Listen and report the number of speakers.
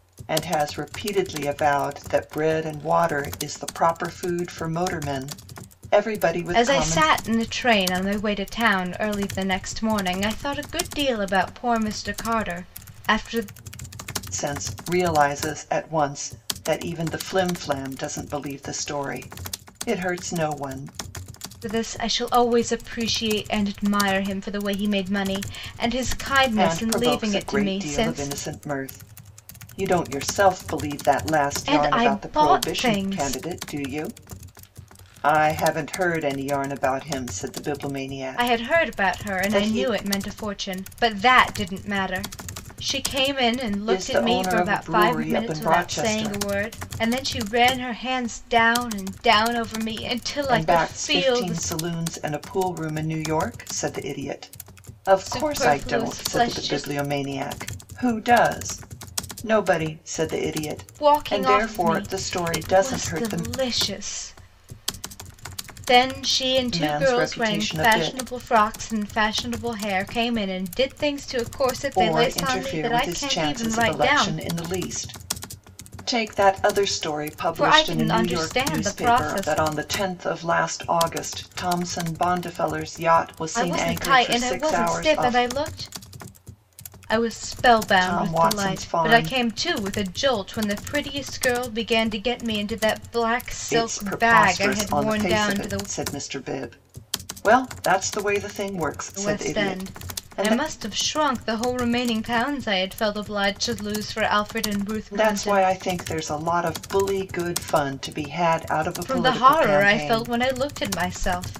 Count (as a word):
two